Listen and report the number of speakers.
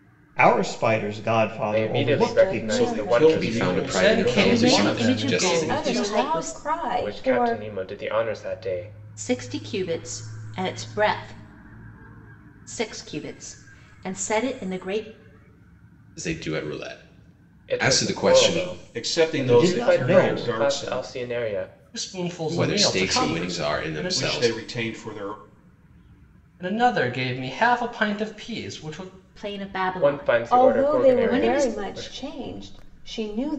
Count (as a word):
seven